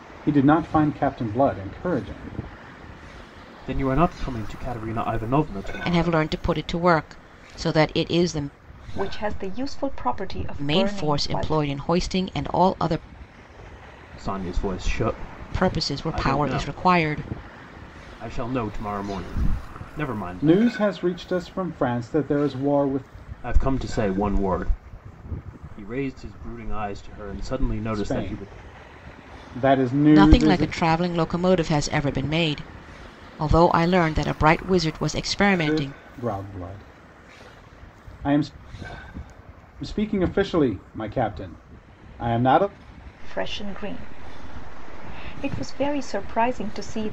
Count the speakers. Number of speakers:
four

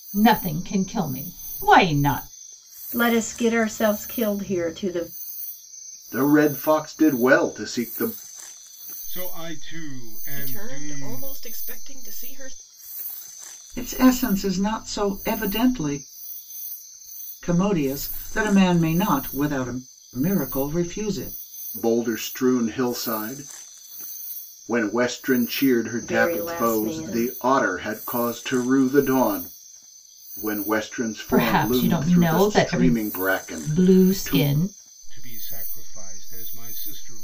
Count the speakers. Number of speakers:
six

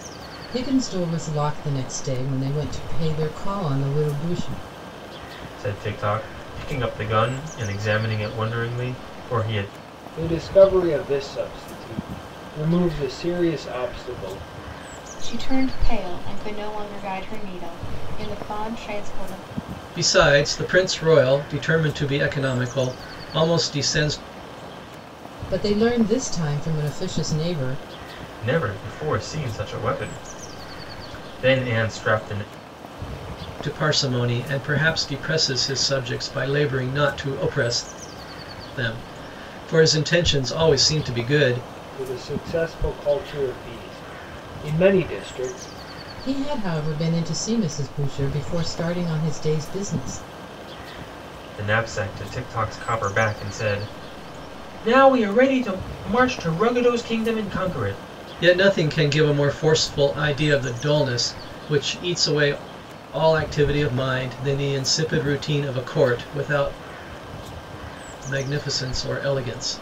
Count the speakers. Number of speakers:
five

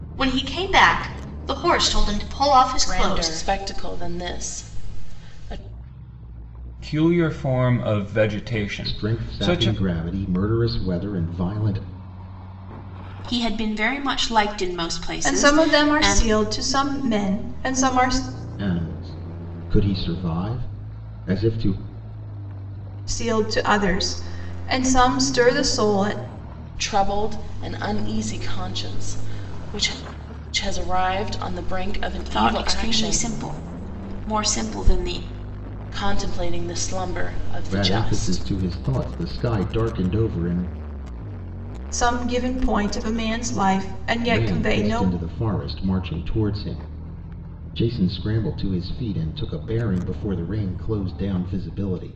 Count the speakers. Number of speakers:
six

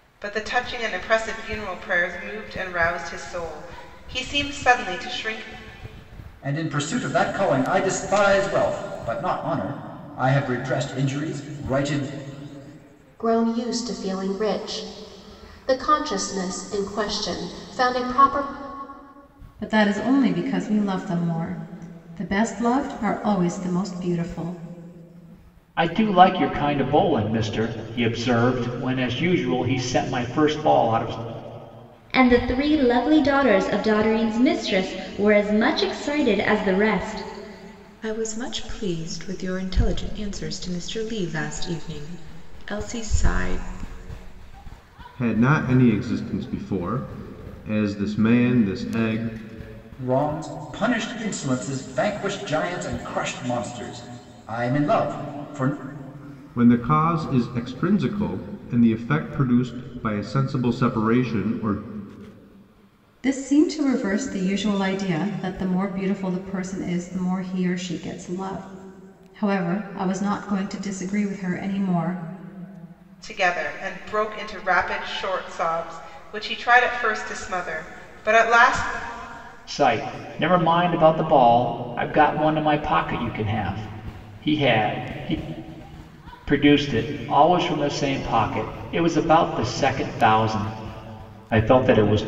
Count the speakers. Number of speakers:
eight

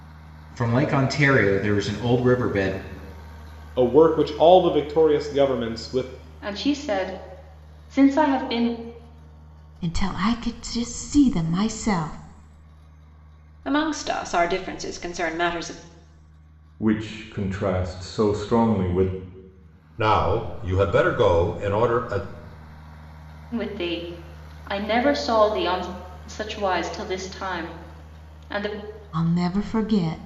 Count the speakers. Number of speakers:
seven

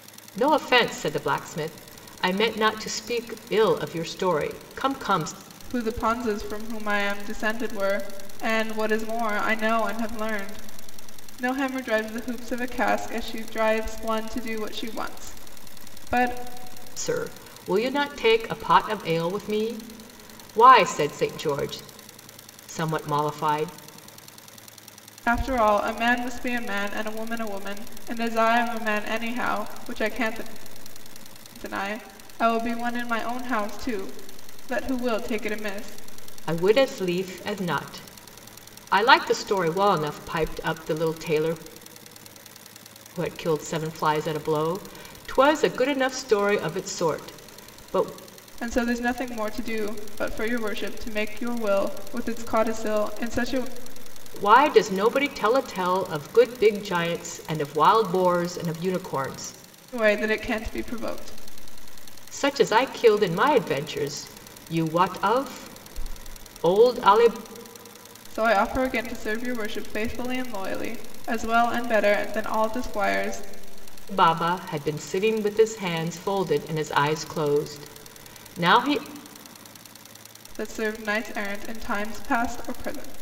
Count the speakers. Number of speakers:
two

